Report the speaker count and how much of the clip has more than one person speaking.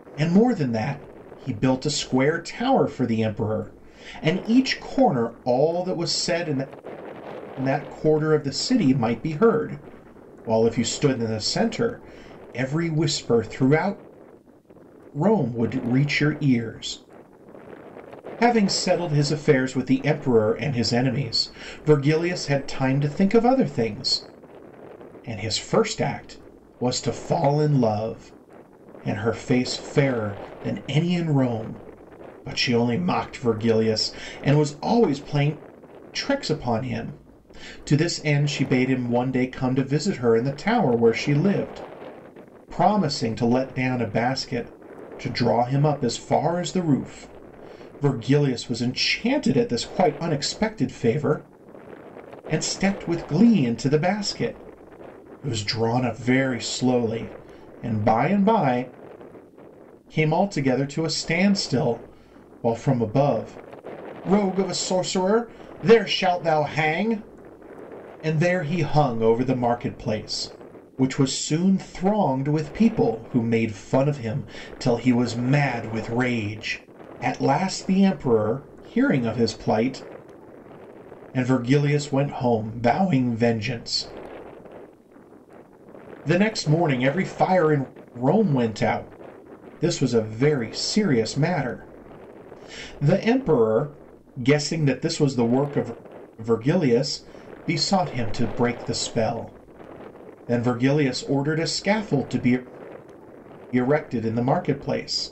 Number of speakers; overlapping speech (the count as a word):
one, no overlap